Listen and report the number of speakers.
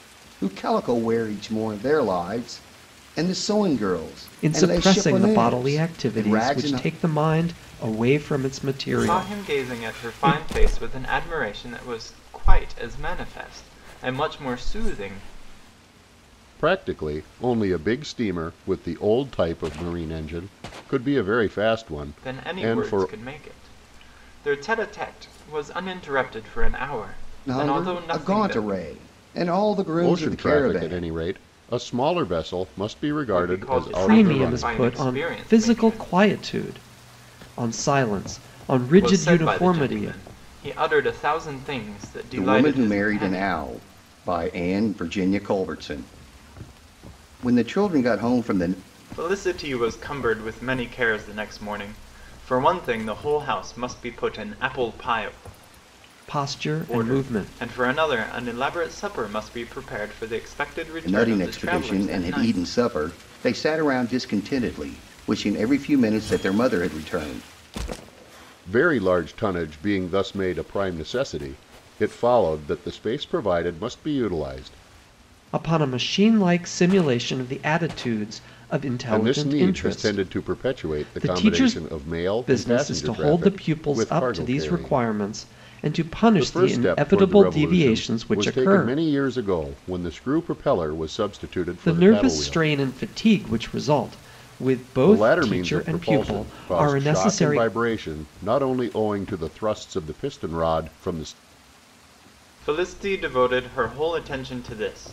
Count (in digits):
4